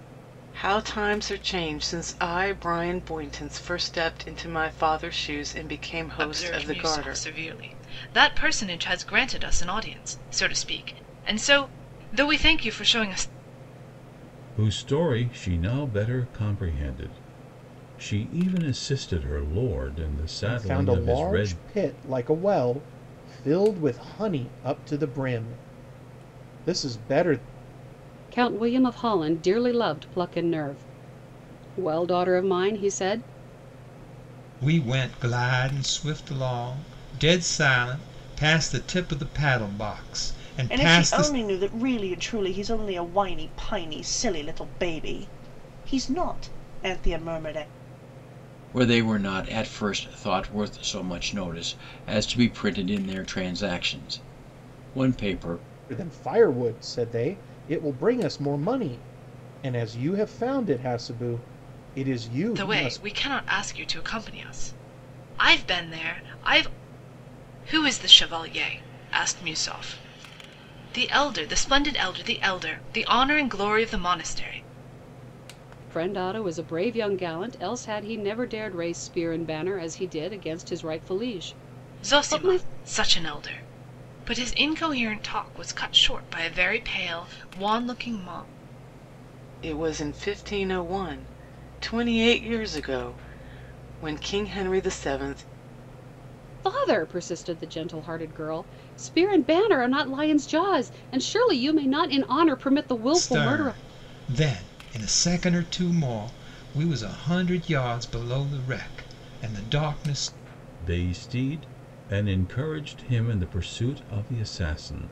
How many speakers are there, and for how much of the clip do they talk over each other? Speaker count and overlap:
8, about 4%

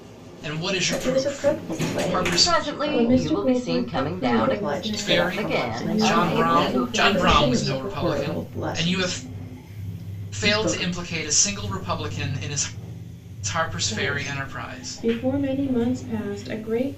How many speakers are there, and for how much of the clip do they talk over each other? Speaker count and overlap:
4, about 61%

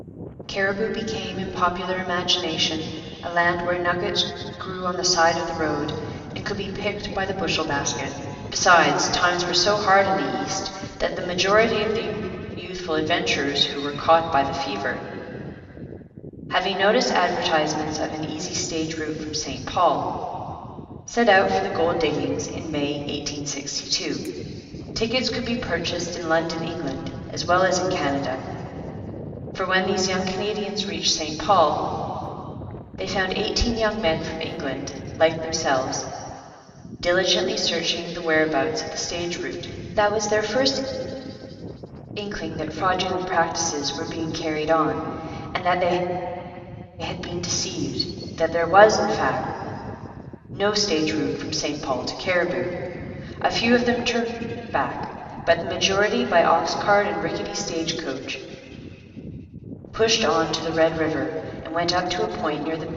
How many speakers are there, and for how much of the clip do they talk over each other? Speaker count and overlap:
1, no overlap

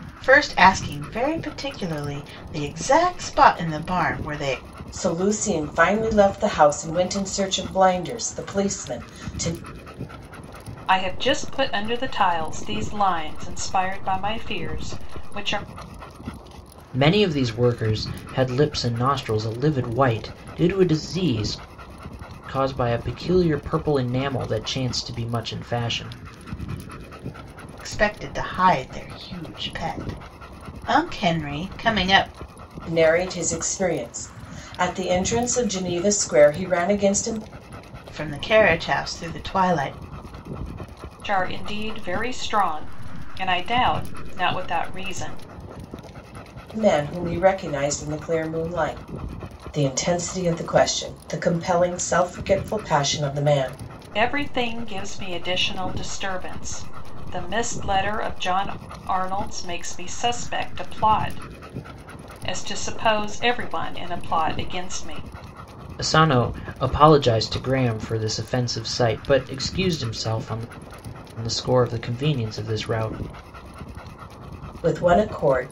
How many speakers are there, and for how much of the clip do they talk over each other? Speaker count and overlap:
4, no overlap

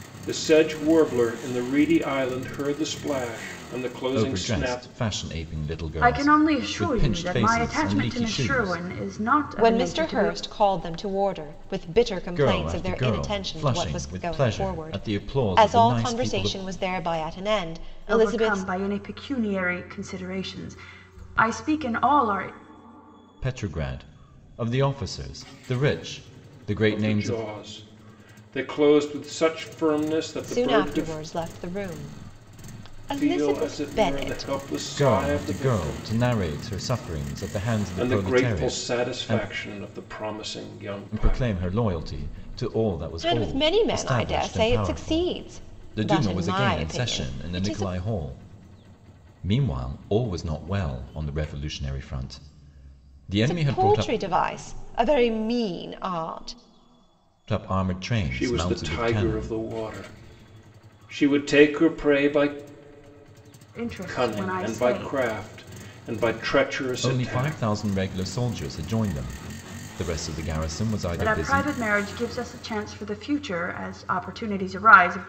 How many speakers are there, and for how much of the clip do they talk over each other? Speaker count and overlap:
4, about 32%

